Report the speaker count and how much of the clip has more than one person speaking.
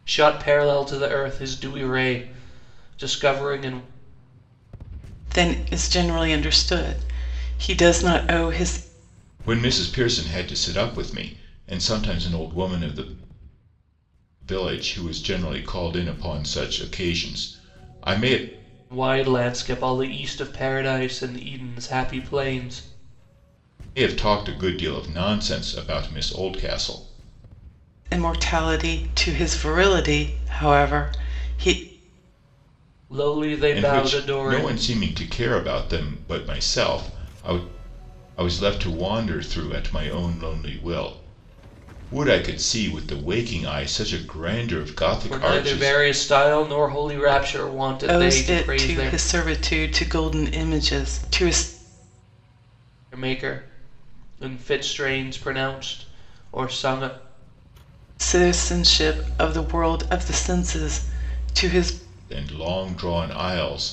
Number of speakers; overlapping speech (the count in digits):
3, about 5%